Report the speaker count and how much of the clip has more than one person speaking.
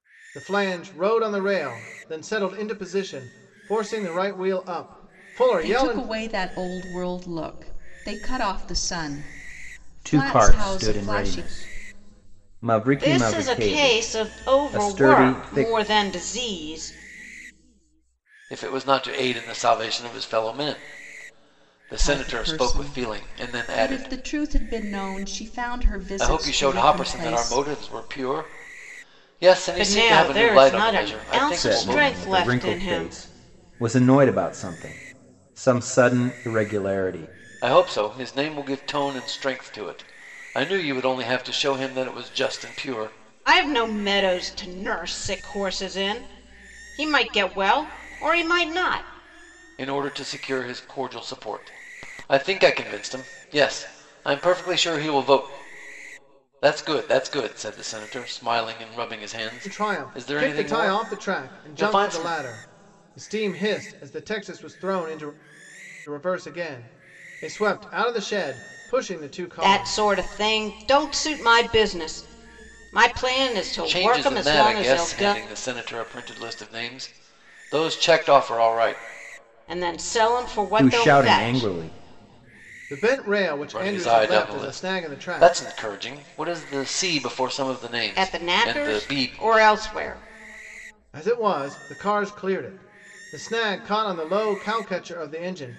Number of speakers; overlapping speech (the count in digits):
5, about 22%